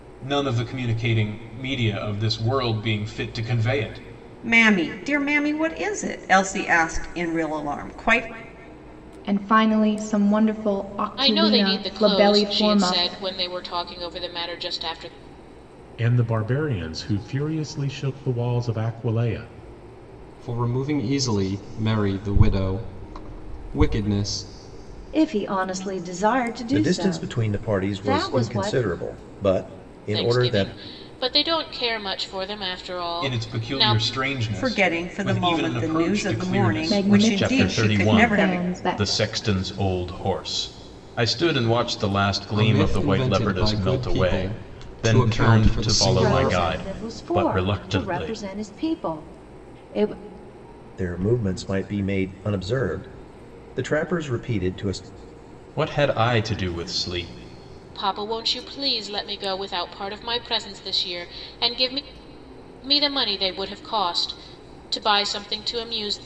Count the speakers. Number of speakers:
eight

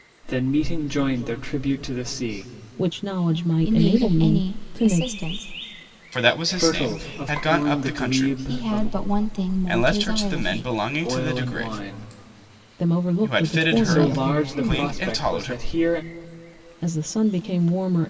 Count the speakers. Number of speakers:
four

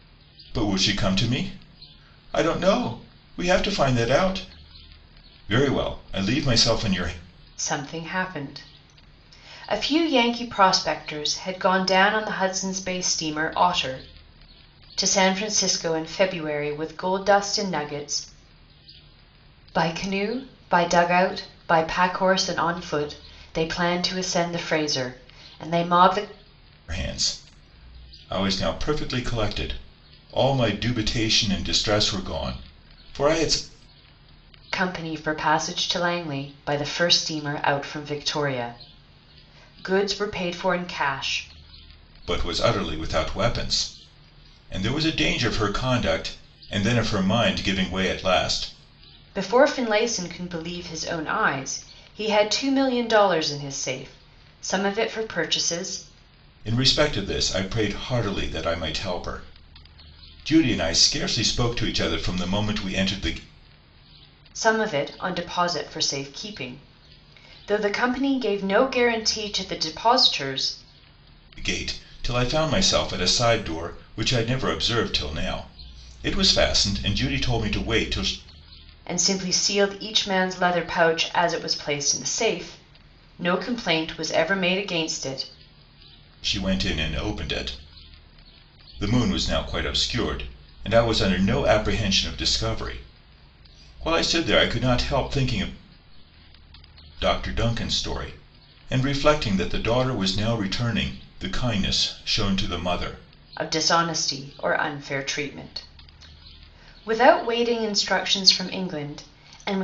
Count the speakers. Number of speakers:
two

